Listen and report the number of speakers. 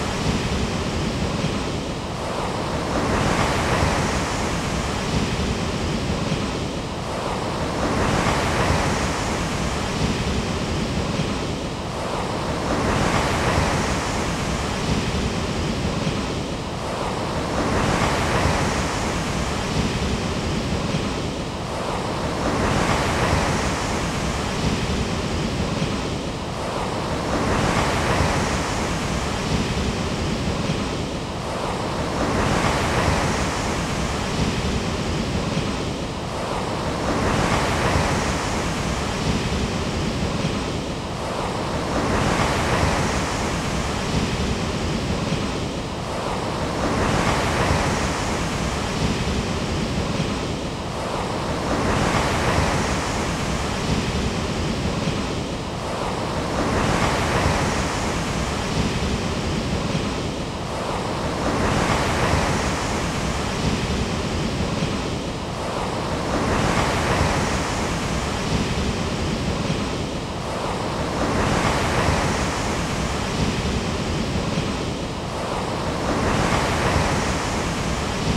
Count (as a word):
zero